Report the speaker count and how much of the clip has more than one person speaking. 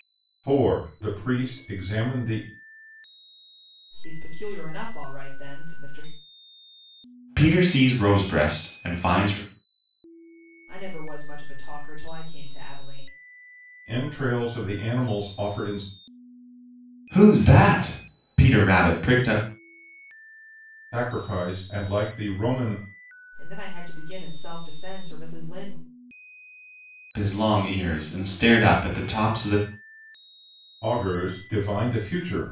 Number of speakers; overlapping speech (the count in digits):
3, no overlap